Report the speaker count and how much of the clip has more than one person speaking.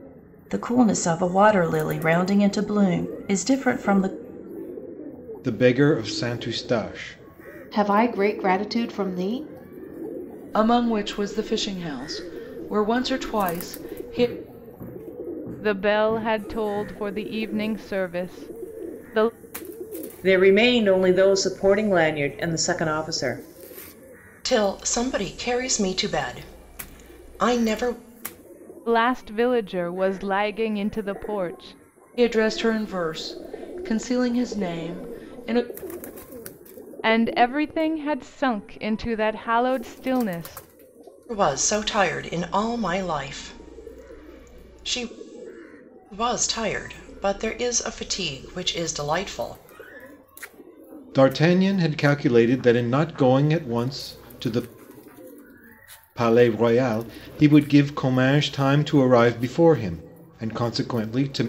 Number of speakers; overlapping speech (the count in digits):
7, no overlap